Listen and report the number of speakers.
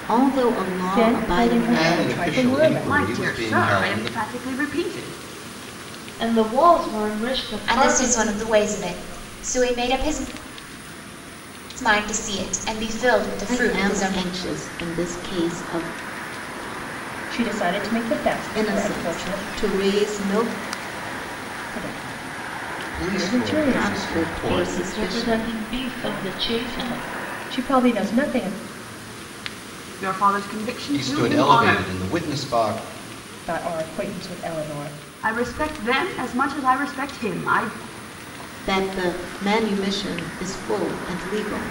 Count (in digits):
6